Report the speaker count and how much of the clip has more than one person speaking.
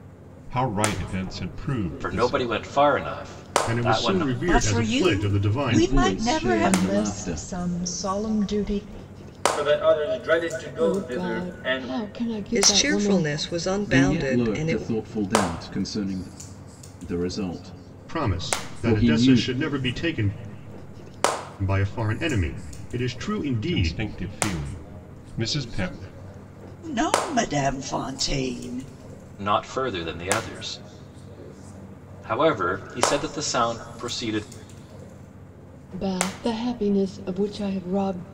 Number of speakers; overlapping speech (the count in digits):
9, about 23%